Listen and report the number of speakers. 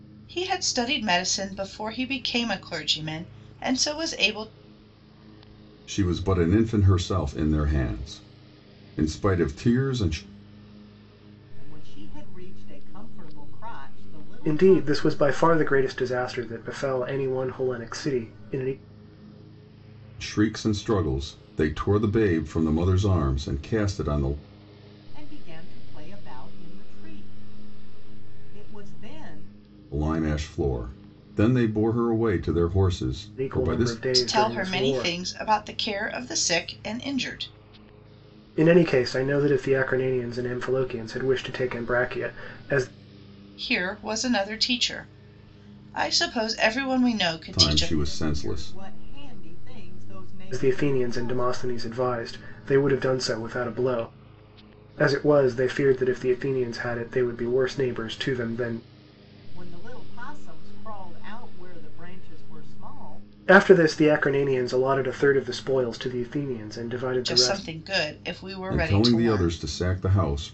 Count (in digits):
4